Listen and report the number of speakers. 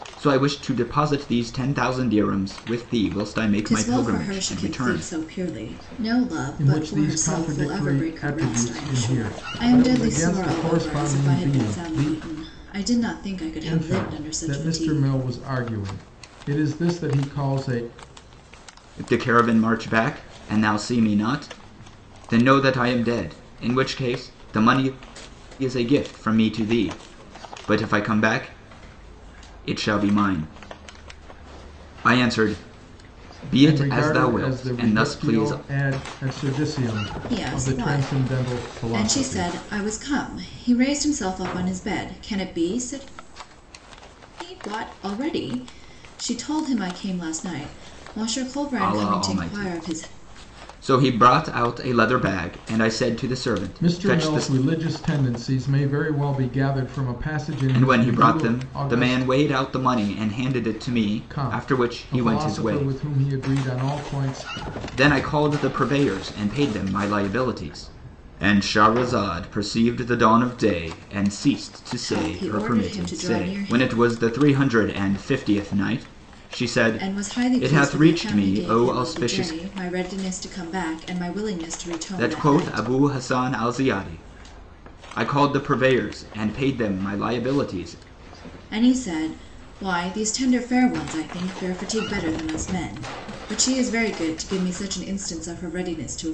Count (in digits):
3